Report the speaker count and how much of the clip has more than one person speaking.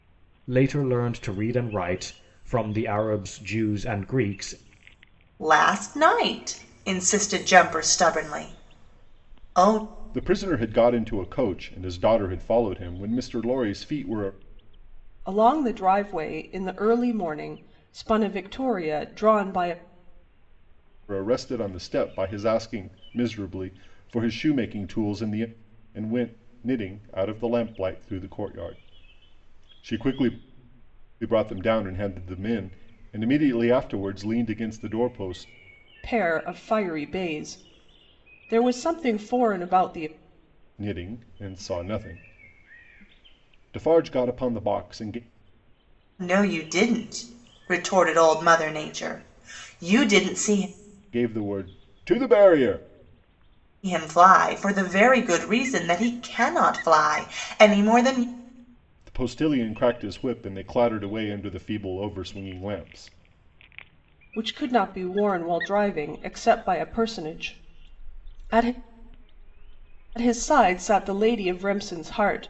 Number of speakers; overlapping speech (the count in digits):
4, no overlap